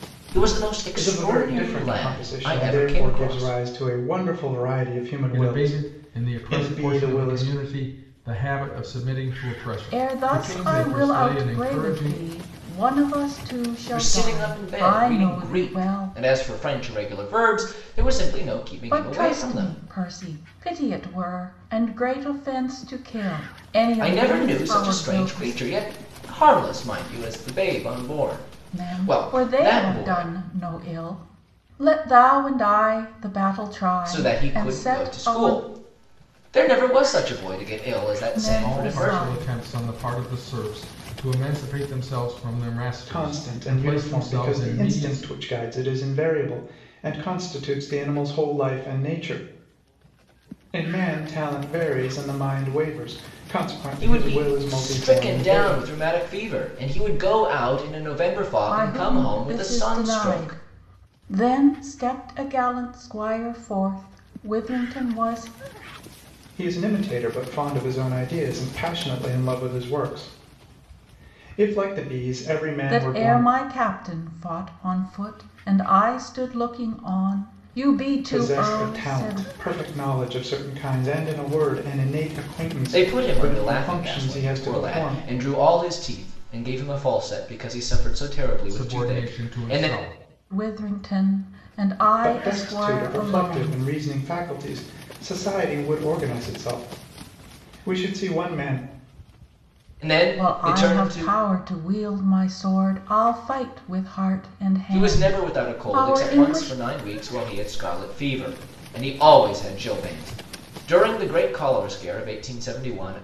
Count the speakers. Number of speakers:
4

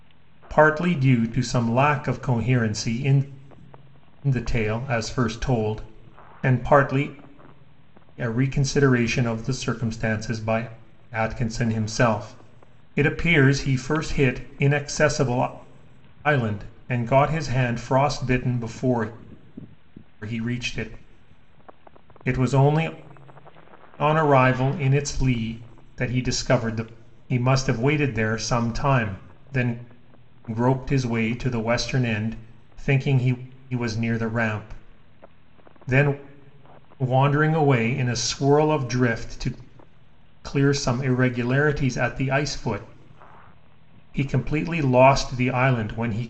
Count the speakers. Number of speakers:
1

